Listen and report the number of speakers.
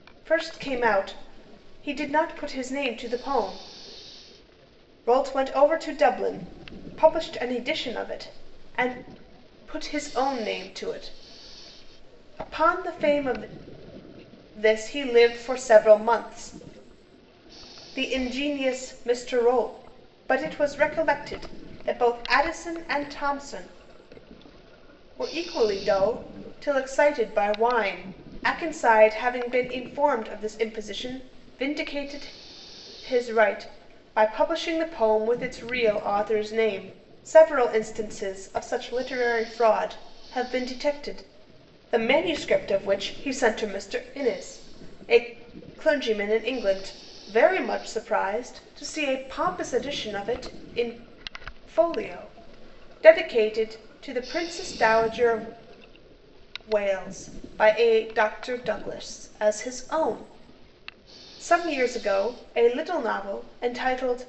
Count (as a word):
one